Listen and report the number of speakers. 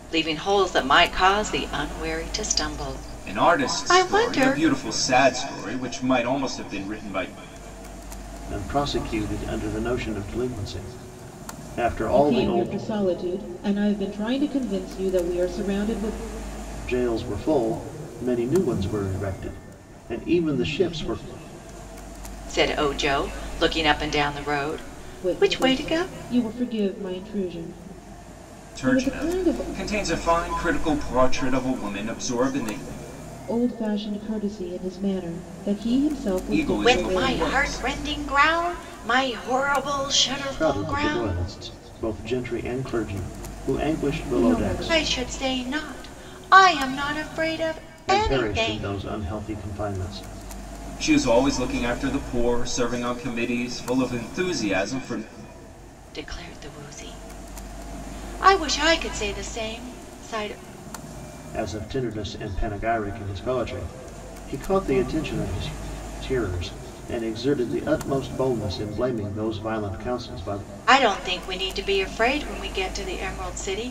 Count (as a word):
four